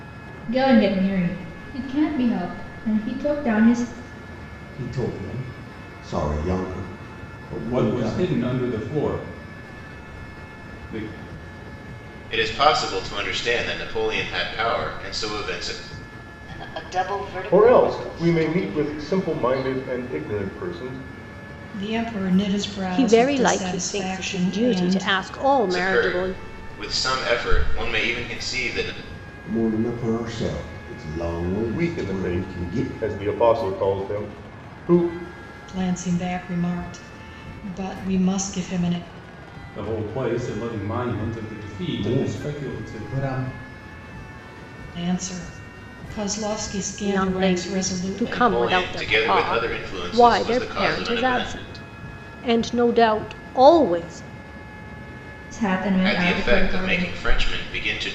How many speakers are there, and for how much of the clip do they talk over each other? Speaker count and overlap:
8, about 24%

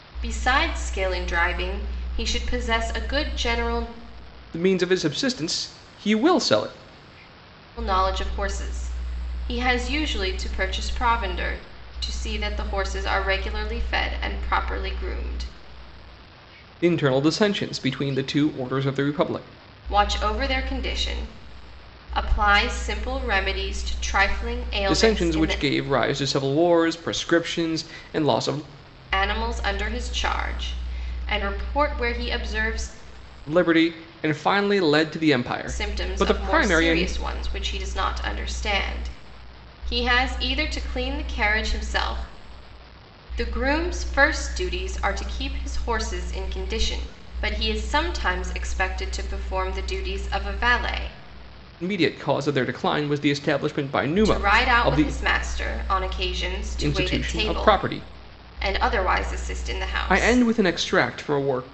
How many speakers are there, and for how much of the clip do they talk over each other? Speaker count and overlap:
2, about 7%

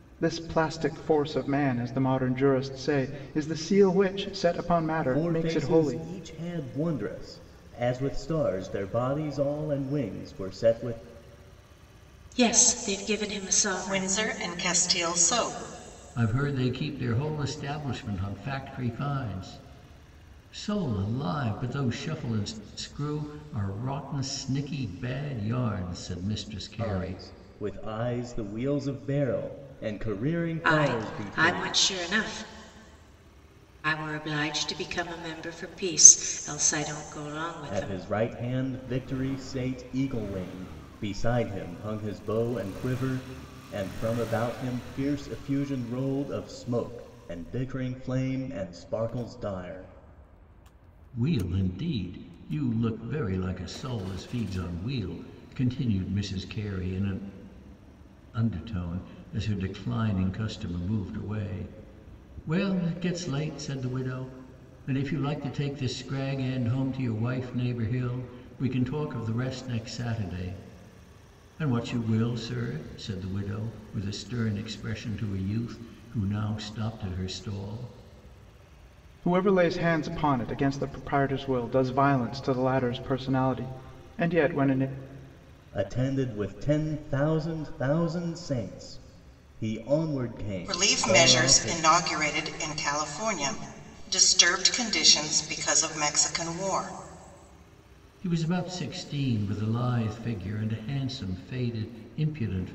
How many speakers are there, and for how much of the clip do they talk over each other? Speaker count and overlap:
5, about 4%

